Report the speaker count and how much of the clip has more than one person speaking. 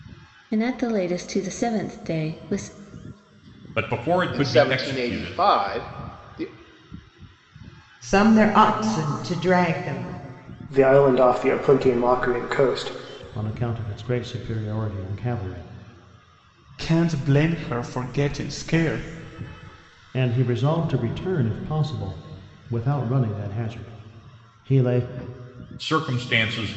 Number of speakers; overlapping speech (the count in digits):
7, about 4%